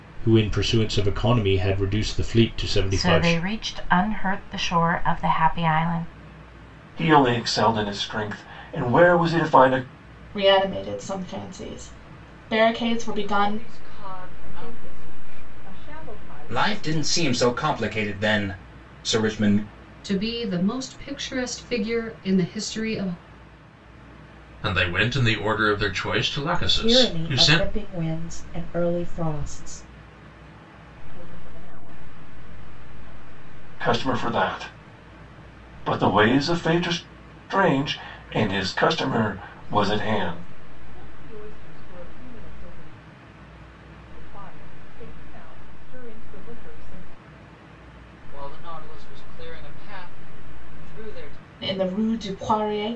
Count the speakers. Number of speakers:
ten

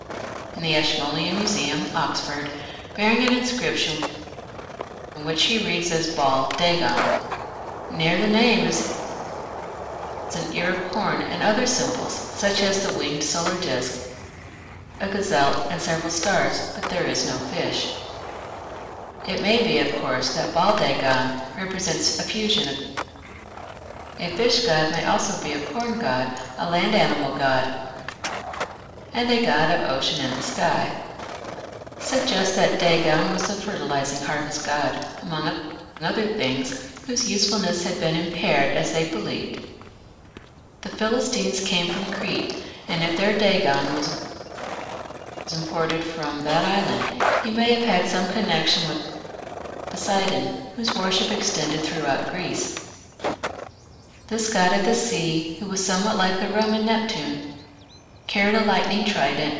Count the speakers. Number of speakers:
one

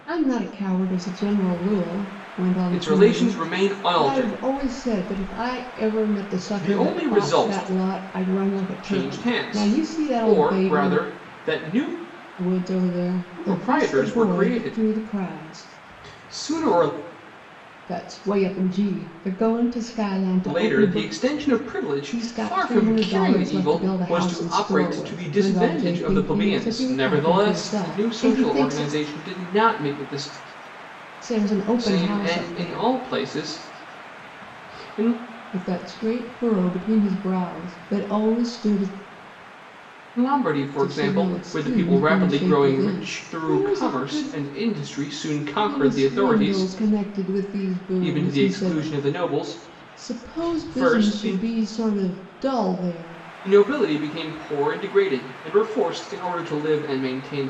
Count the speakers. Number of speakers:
two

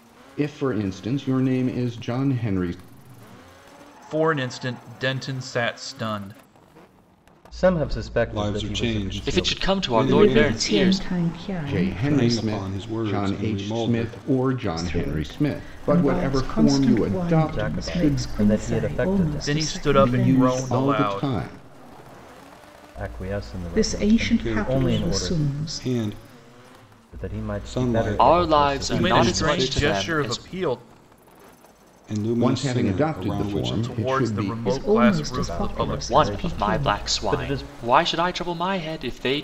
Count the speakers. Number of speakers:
six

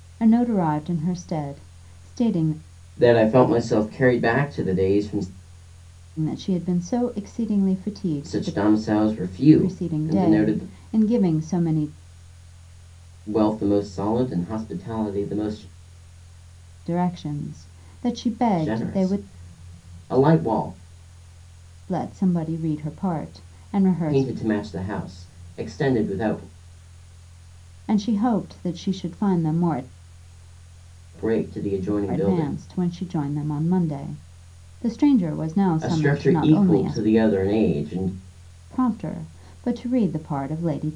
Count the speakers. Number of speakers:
two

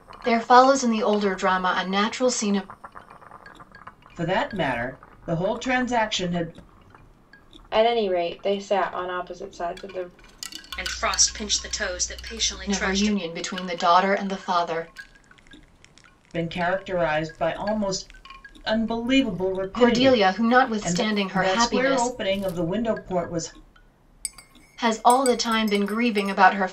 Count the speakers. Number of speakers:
four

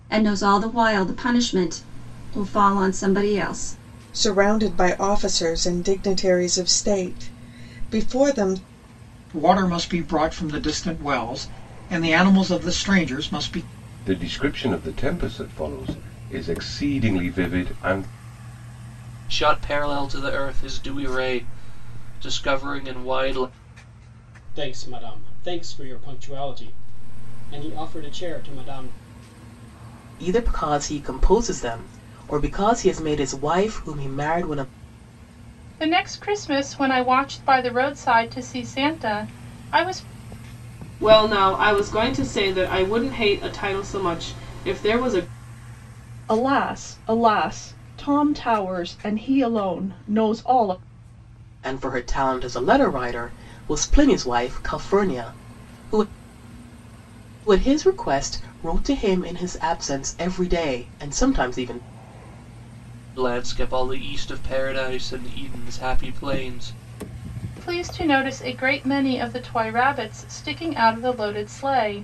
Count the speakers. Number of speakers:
ten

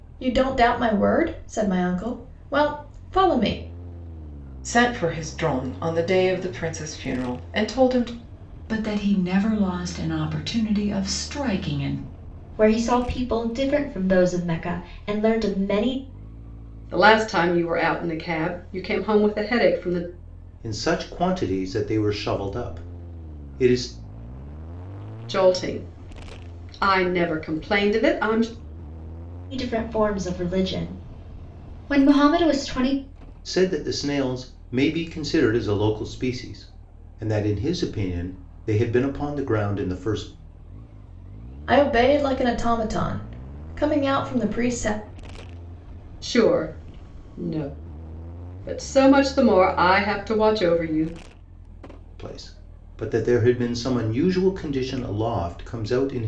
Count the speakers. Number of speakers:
six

